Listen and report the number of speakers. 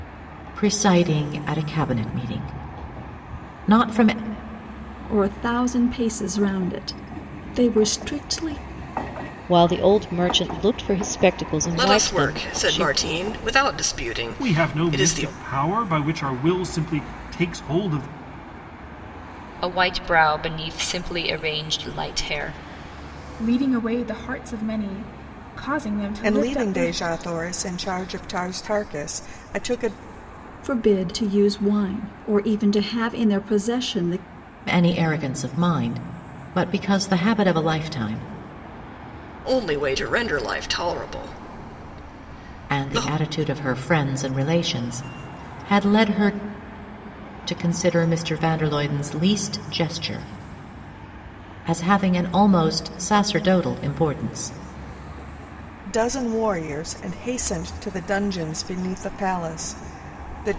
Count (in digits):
8